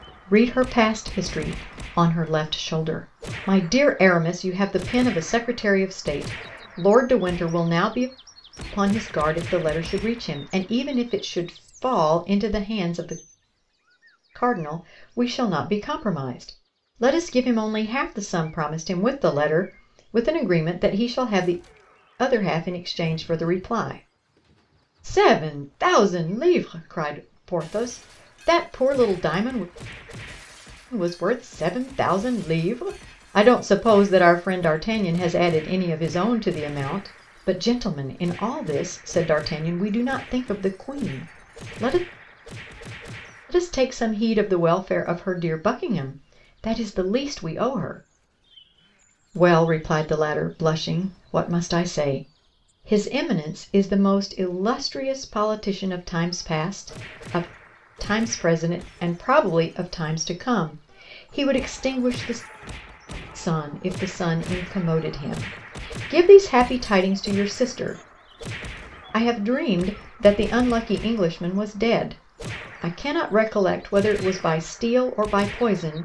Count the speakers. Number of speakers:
1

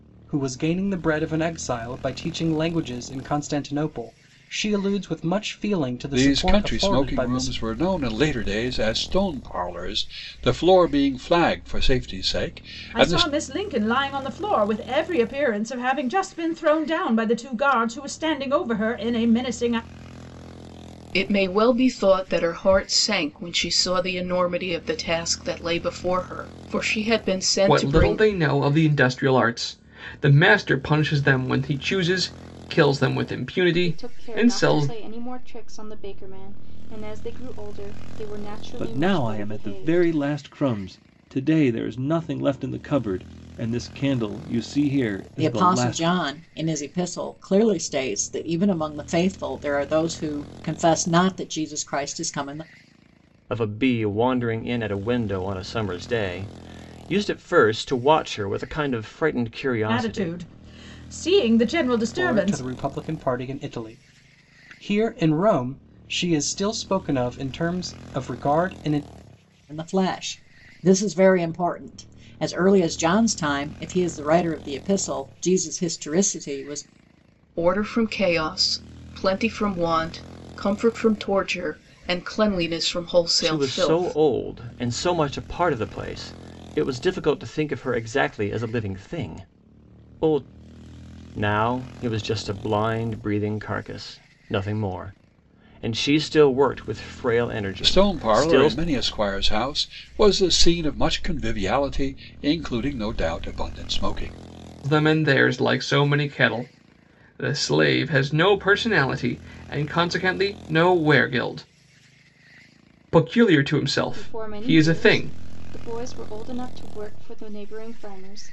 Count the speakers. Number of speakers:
9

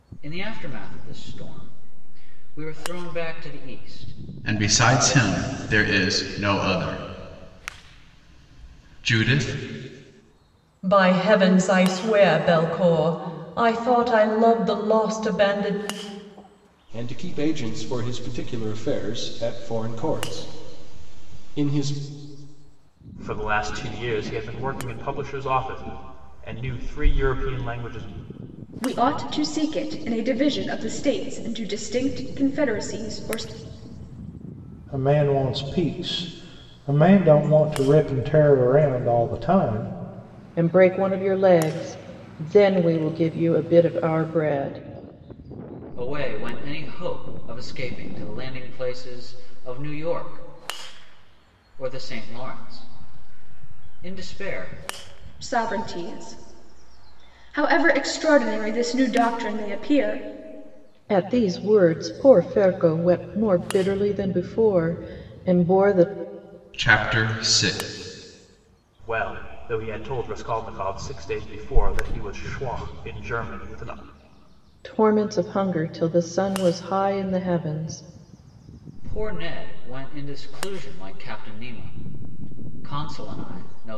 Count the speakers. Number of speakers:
8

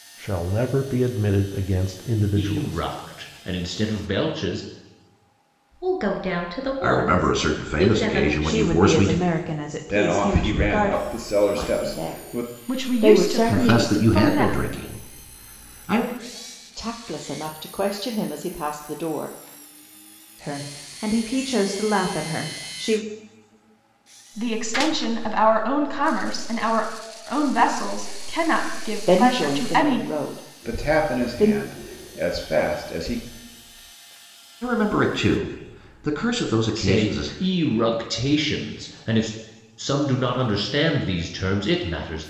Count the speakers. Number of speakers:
8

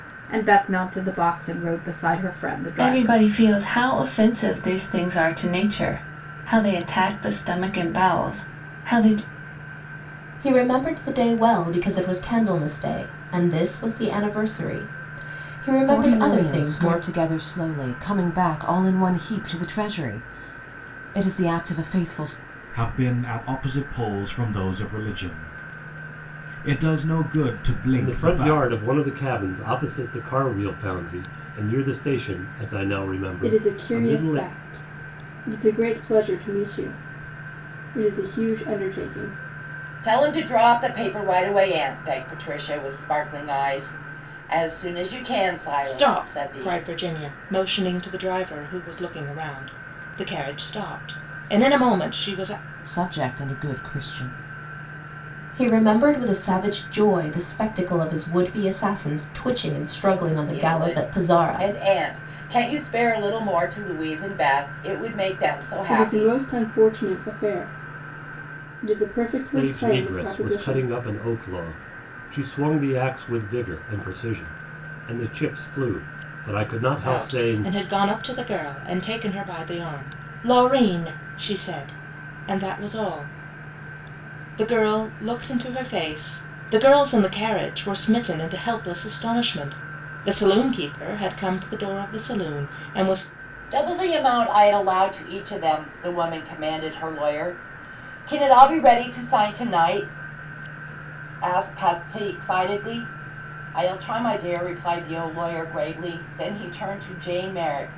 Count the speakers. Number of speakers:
9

